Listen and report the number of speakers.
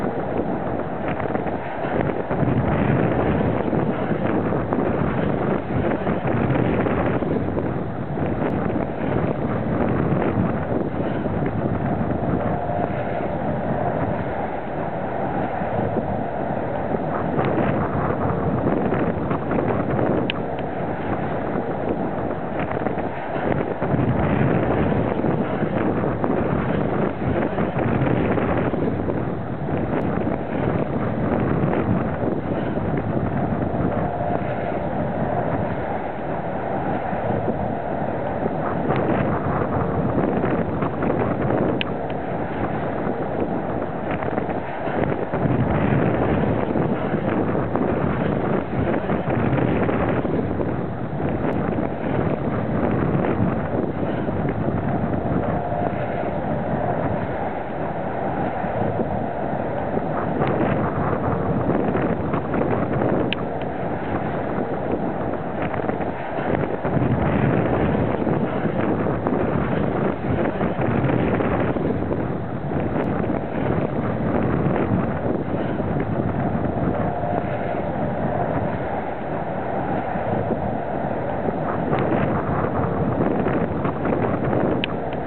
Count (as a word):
zero